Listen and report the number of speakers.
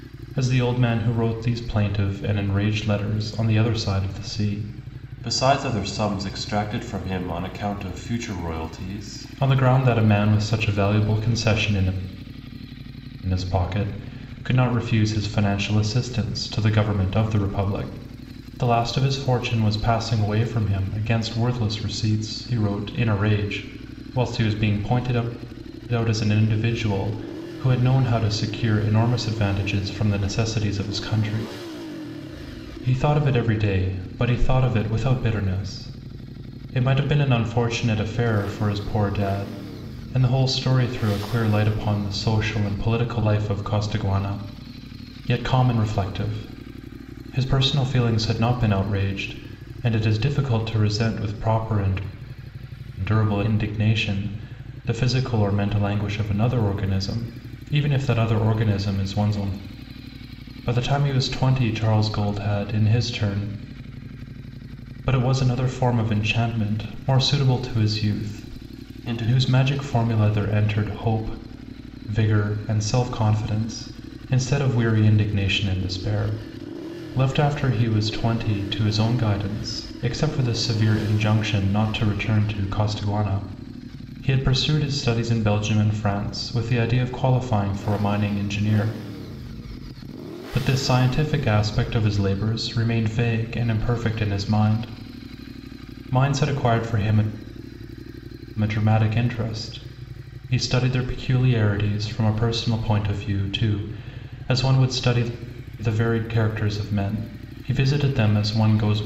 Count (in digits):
1